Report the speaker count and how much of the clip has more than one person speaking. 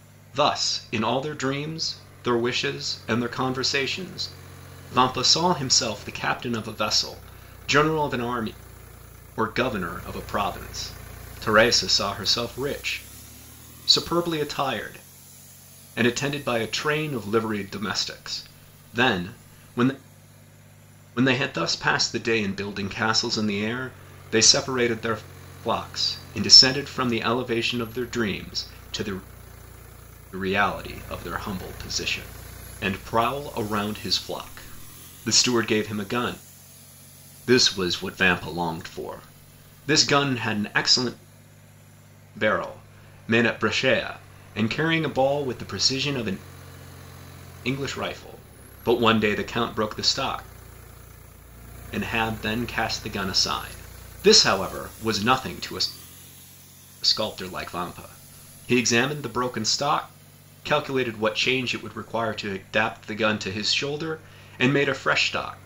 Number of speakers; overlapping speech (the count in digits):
1, no overlap